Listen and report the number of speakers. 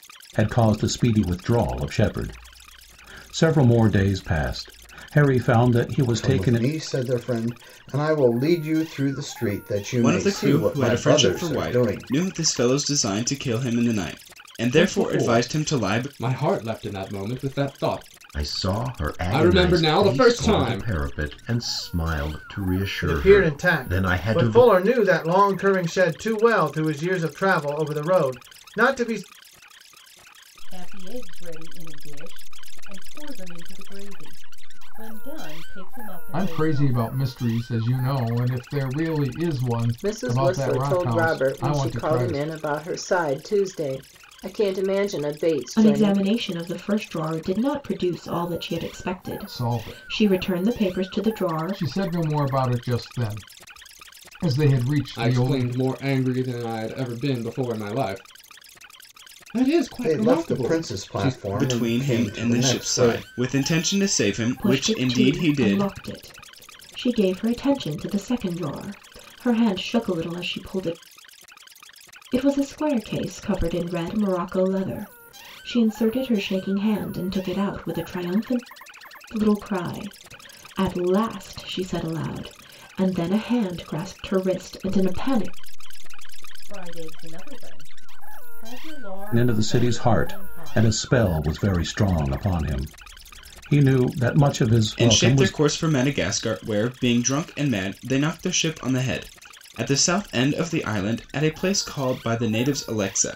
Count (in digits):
10